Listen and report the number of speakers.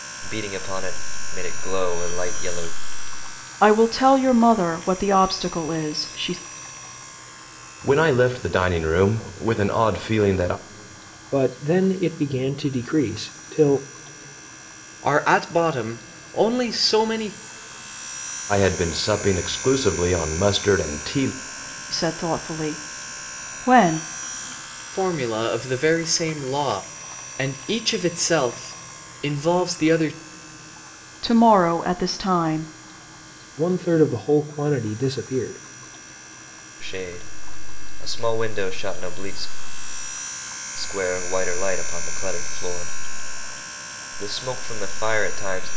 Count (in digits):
5